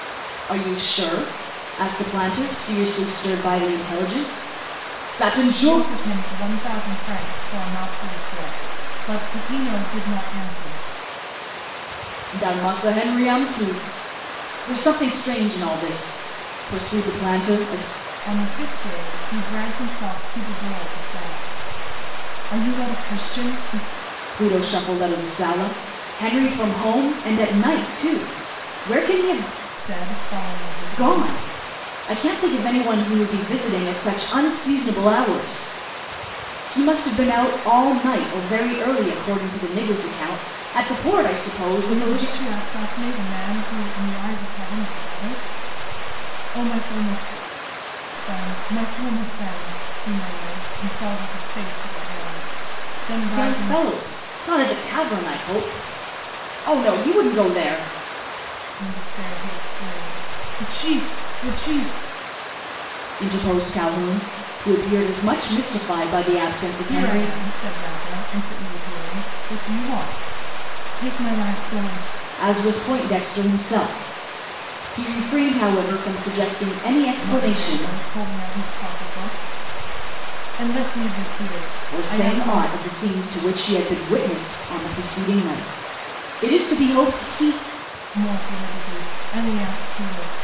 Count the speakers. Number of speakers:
two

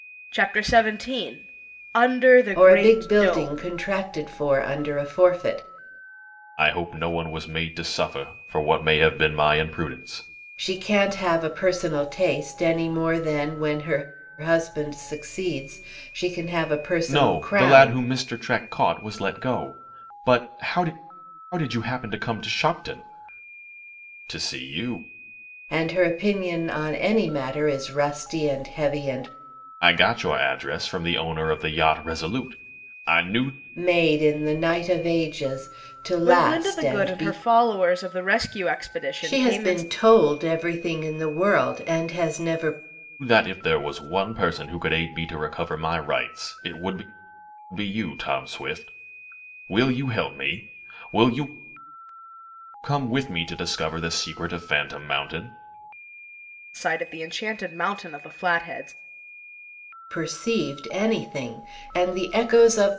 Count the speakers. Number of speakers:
three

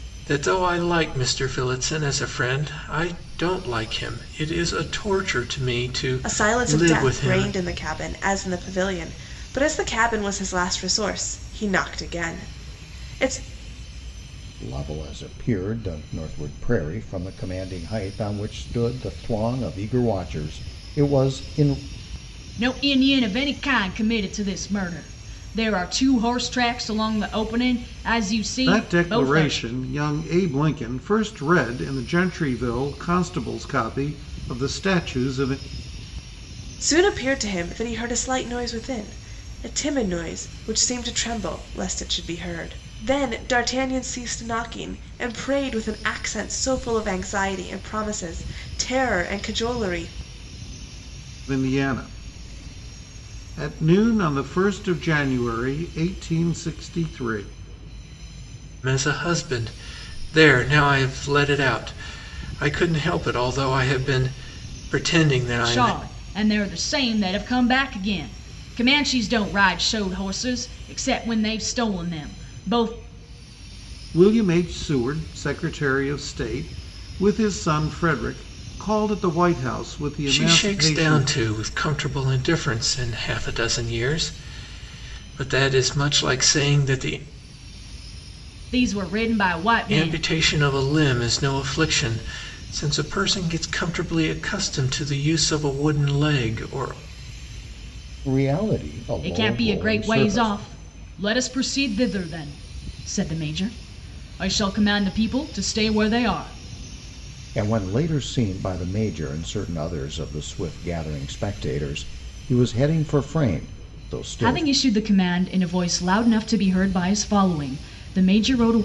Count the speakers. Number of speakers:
five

